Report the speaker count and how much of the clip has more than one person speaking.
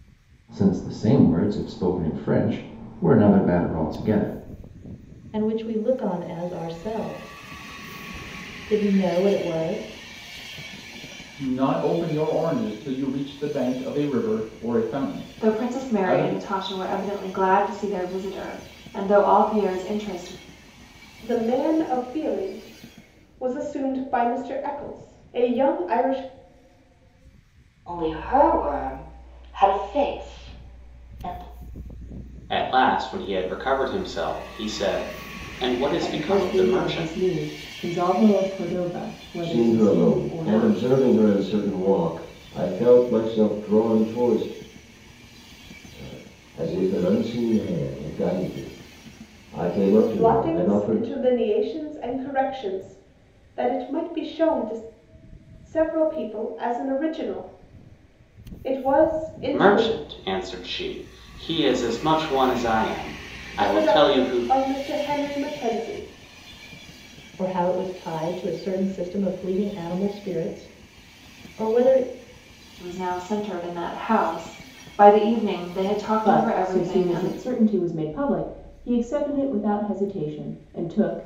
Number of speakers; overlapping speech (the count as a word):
nine, about 10%